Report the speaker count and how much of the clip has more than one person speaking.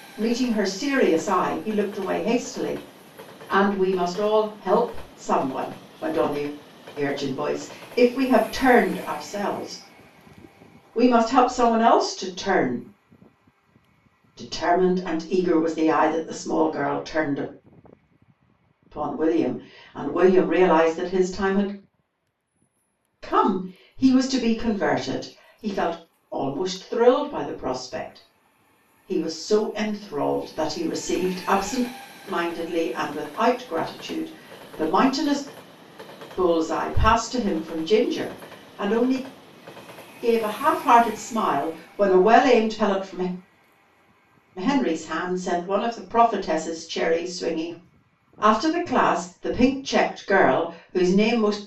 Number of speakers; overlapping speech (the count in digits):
1, no overlap